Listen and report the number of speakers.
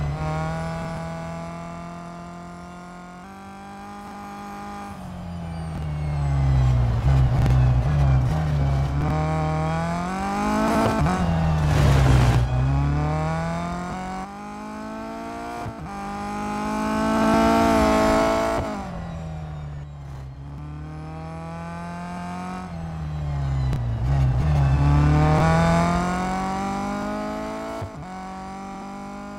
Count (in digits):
0